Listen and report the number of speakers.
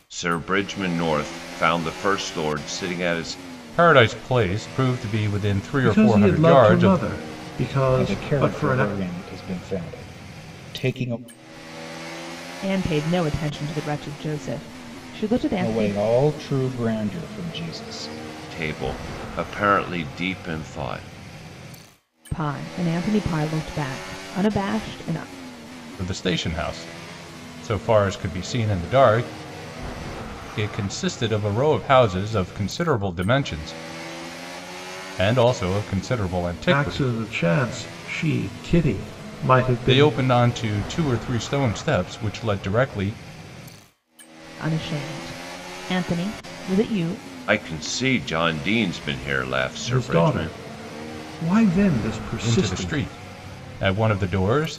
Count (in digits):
5